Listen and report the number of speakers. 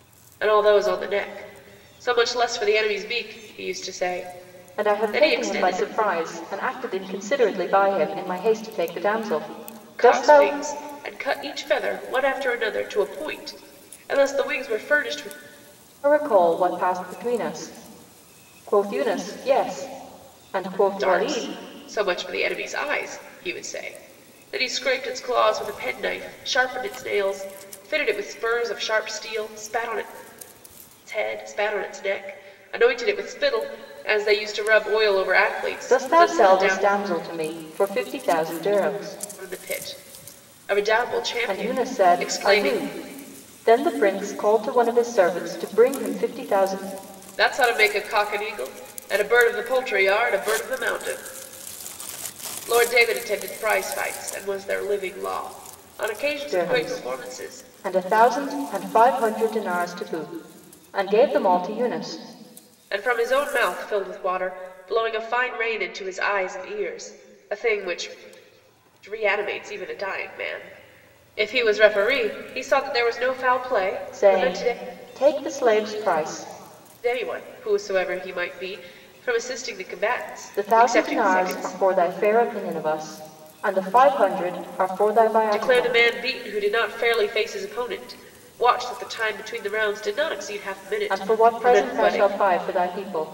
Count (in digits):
2